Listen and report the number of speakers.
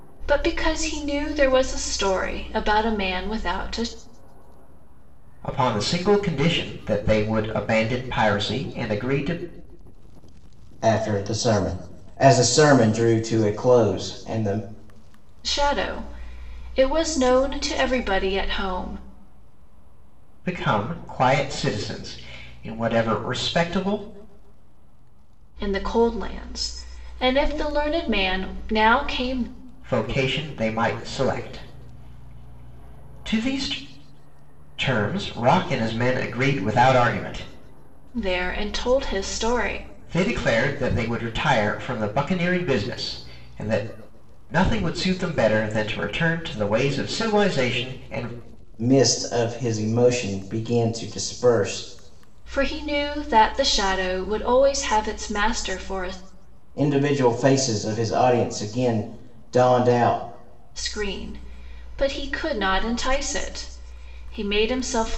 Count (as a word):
three